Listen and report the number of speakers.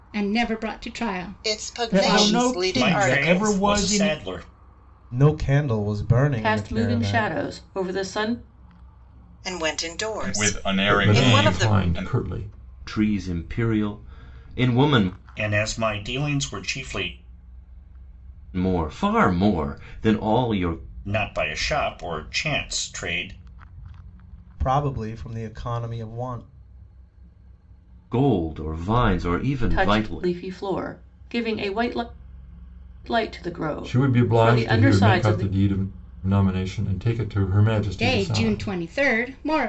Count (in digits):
10